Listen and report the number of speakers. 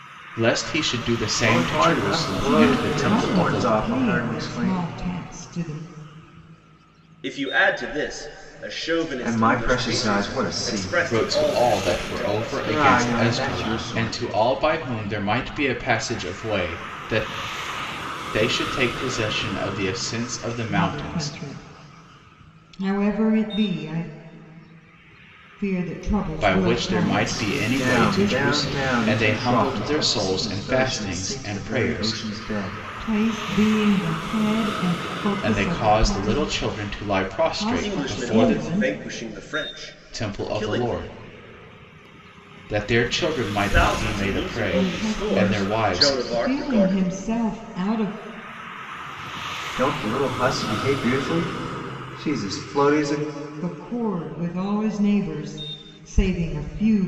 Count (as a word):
four